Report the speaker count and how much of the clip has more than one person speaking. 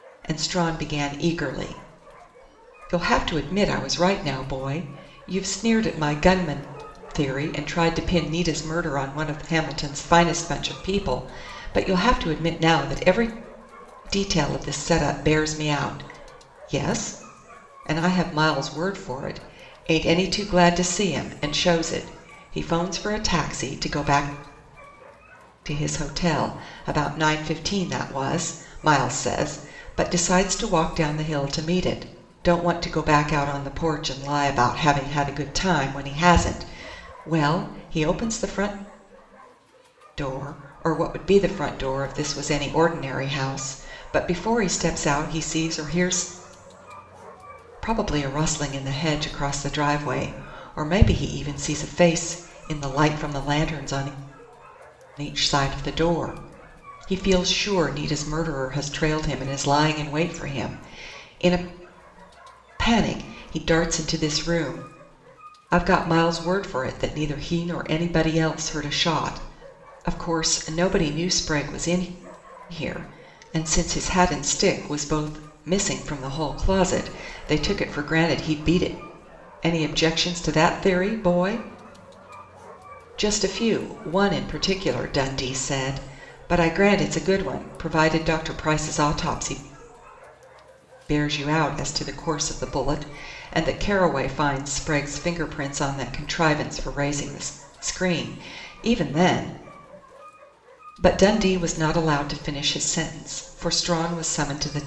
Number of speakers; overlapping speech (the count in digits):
1, no overlap